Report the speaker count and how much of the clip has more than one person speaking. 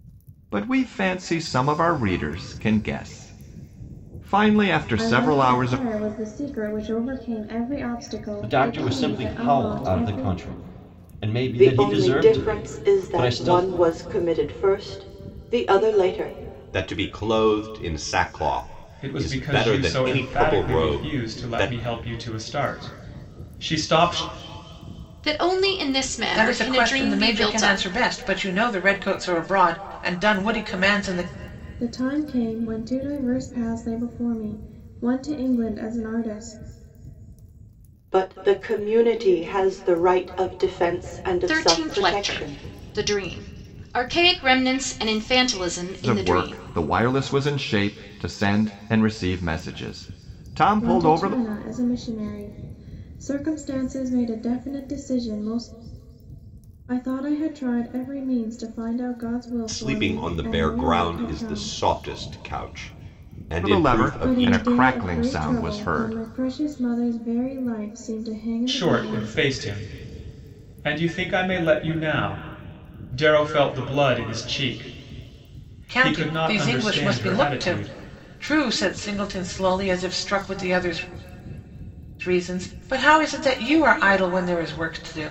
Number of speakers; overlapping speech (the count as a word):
eight, about 23%